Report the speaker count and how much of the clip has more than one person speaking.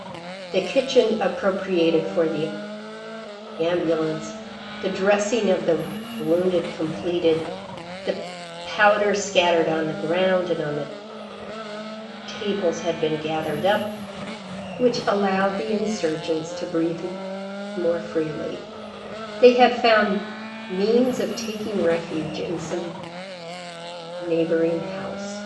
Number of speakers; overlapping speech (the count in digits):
1, no overlap